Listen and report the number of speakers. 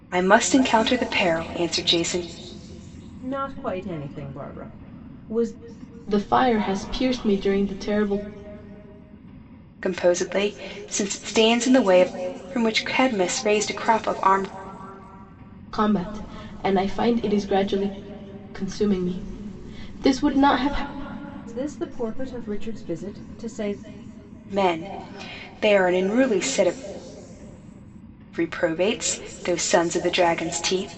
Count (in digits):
3